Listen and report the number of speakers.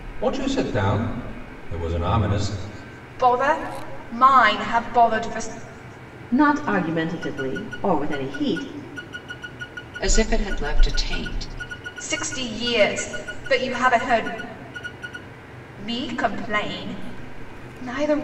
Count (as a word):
four